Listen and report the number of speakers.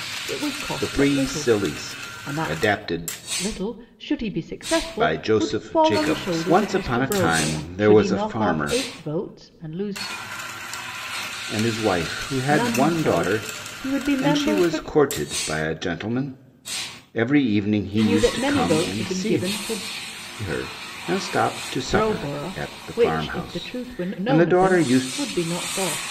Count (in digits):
2